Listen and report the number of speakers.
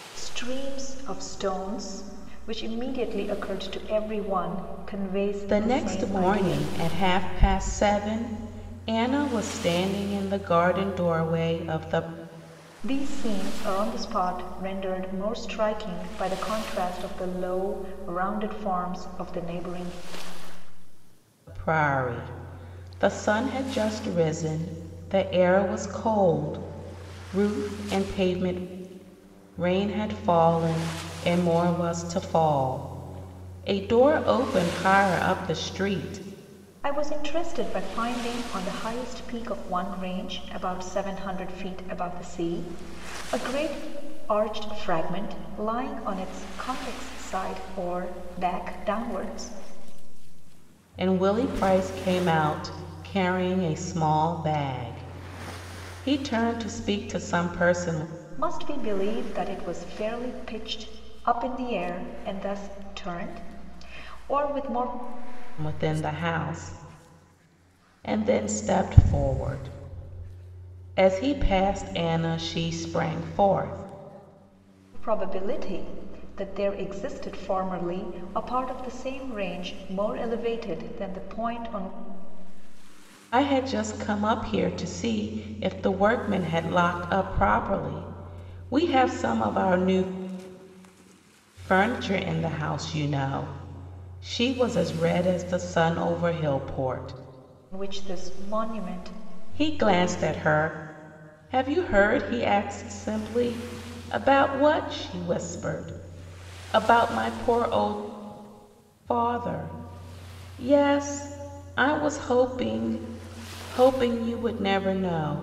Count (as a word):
two